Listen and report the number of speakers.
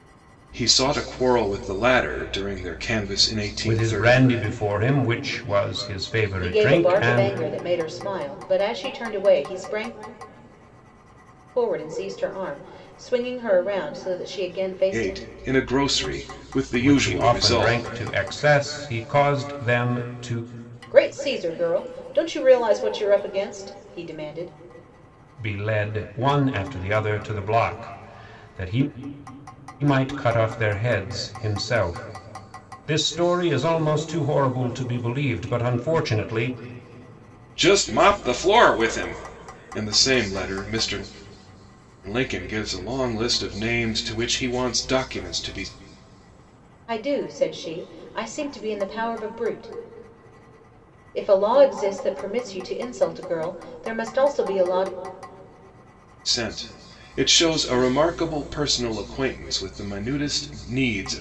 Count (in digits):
3